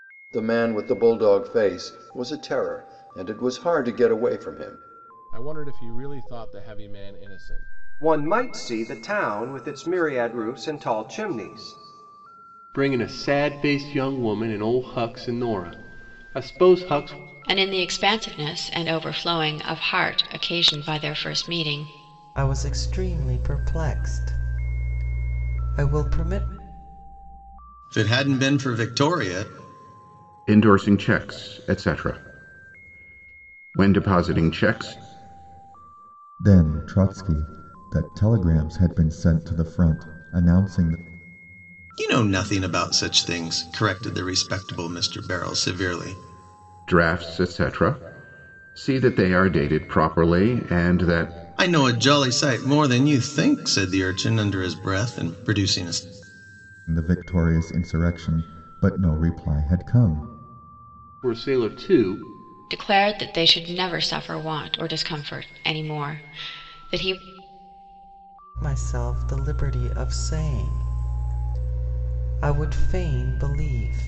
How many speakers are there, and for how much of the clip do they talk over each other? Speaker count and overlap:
9, no overlap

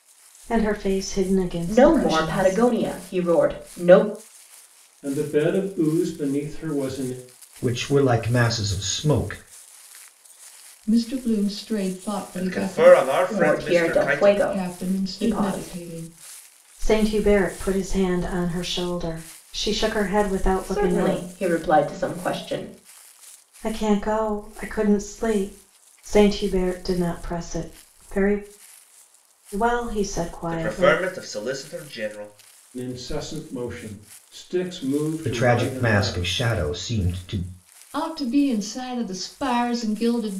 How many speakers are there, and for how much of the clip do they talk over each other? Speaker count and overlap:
6, about 16%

